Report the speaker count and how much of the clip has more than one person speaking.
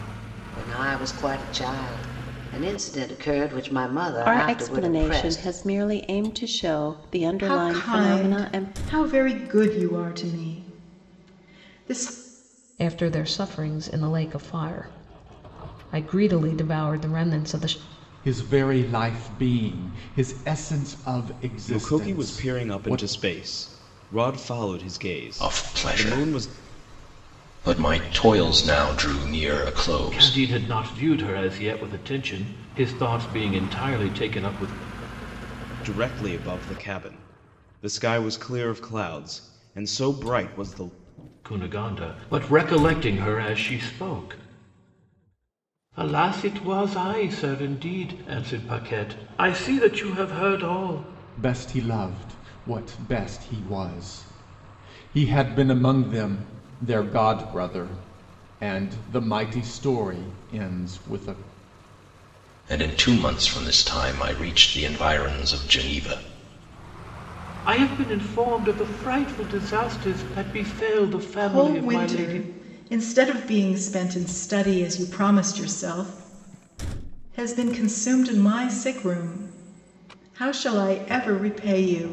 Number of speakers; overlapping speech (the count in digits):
8, about 8%